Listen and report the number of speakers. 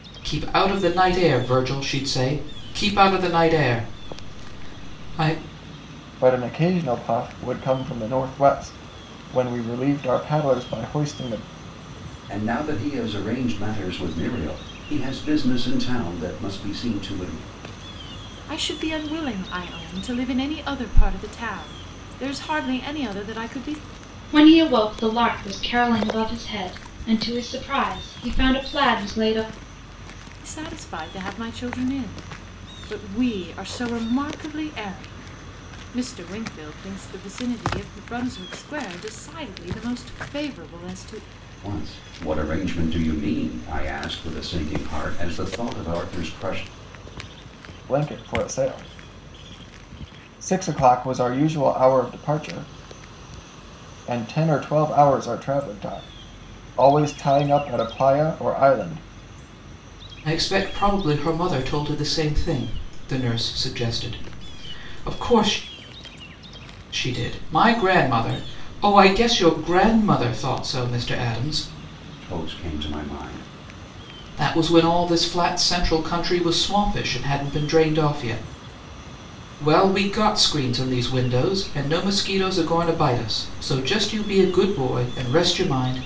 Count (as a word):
five